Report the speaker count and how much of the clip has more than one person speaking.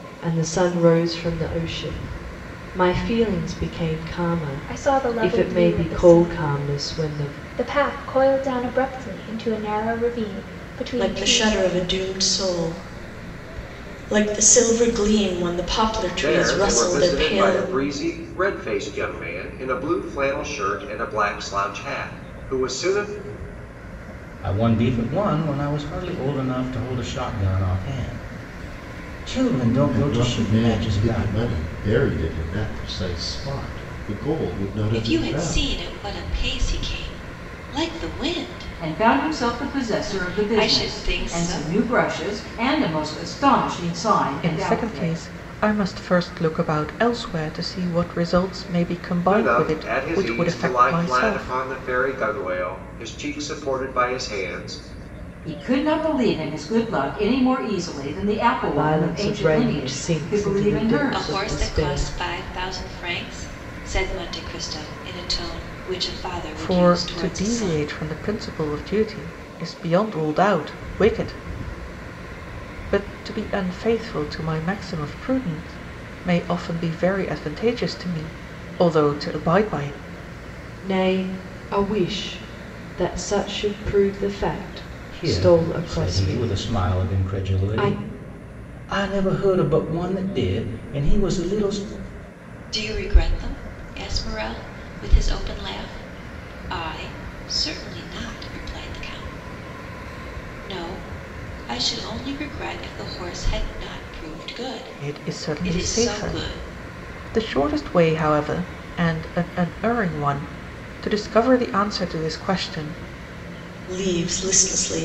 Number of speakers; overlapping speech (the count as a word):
nine, about 20%